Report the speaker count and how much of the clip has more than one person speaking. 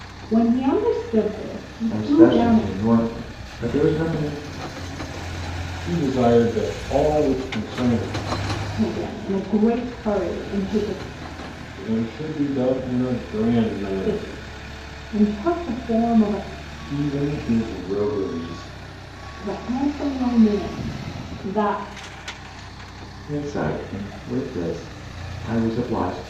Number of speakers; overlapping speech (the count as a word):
three, about 4%